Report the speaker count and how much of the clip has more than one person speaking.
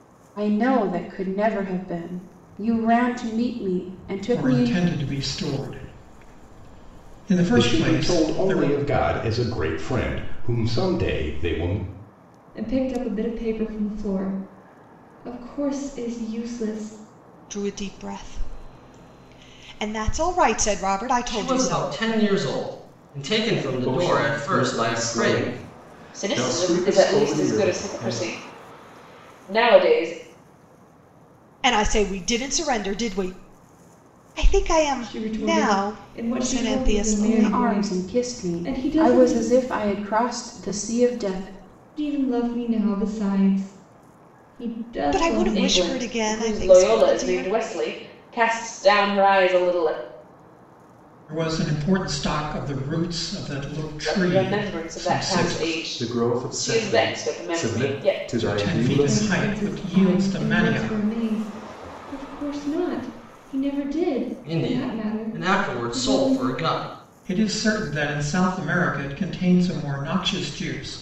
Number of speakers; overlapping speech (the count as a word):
eight, about 31%